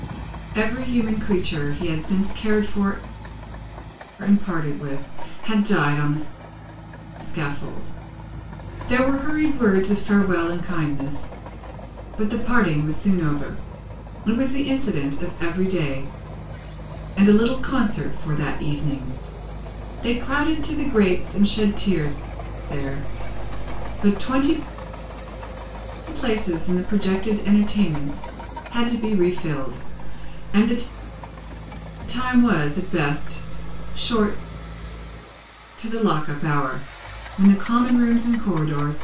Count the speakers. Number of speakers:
one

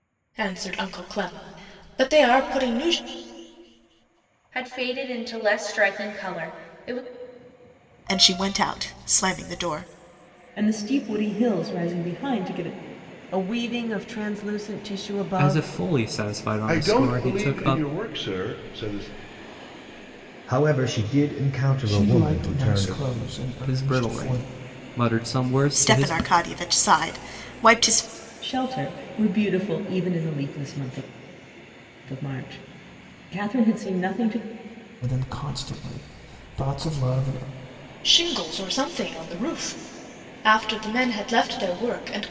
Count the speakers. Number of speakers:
nine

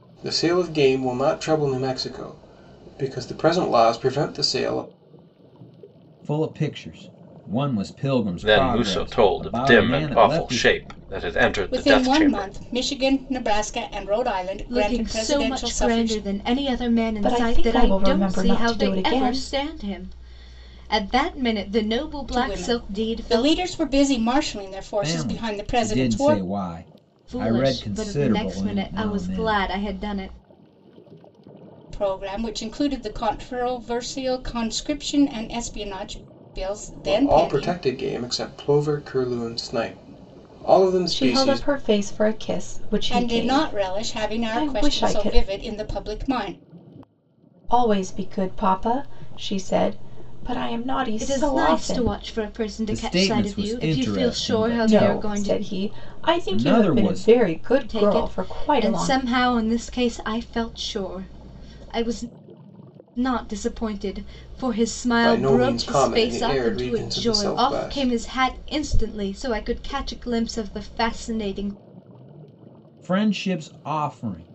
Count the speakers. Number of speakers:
six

